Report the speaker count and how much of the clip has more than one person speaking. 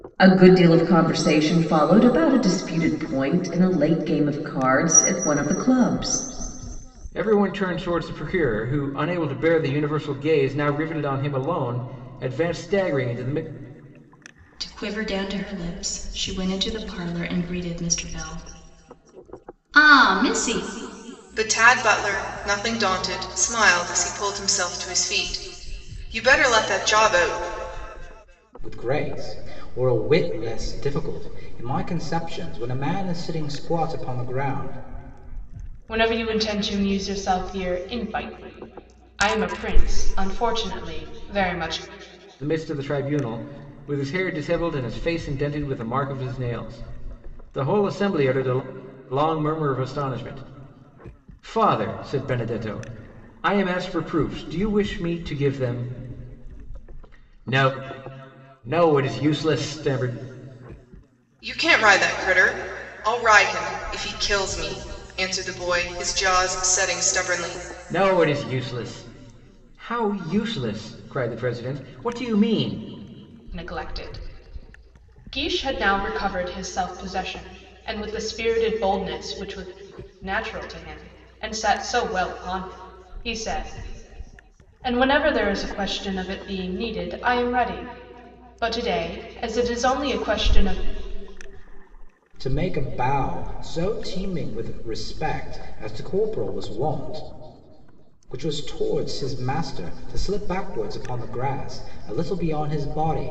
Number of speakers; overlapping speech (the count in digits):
6, no overlap